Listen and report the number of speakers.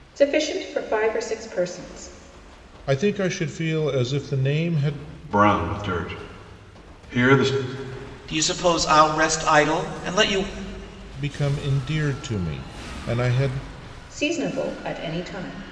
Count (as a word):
four